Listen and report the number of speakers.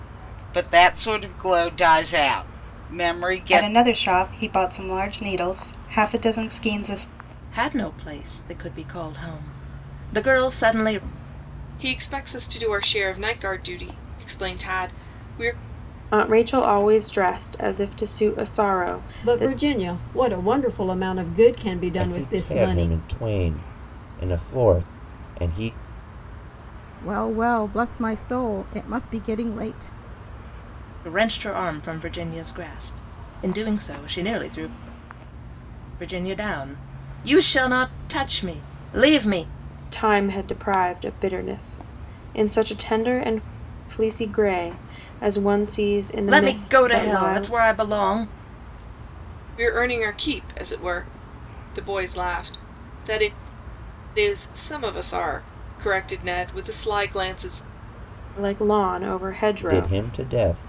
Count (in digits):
8